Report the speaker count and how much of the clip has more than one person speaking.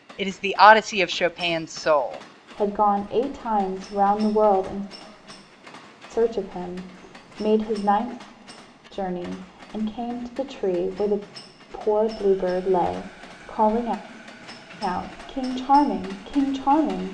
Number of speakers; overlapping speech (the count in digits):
2, no overlap